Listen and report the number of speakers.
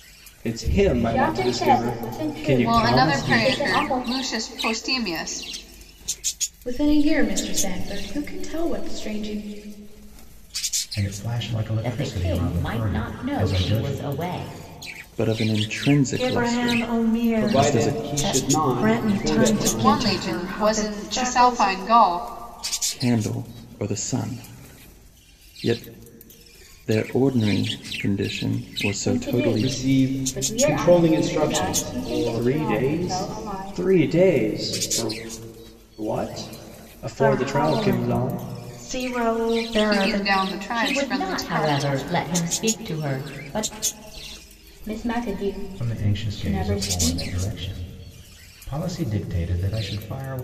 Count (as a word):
nine